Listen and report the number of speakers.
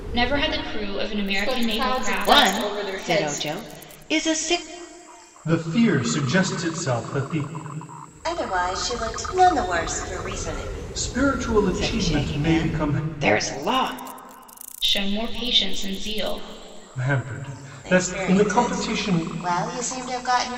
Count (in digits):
5